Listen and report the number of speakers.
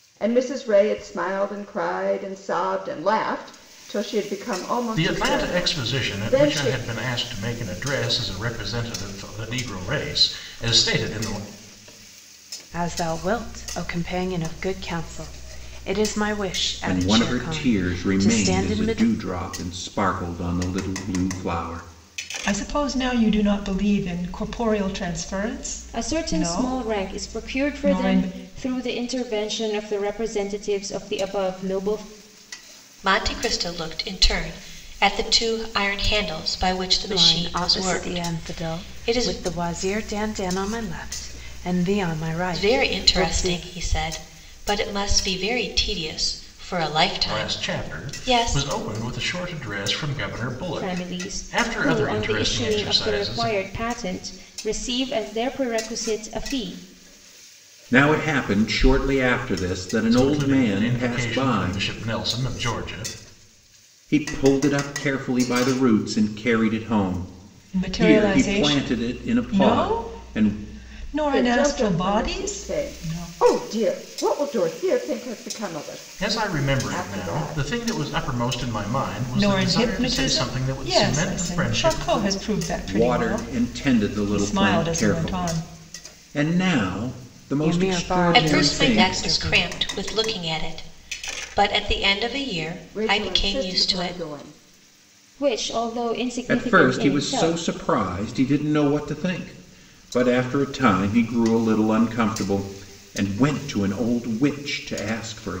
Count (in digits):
7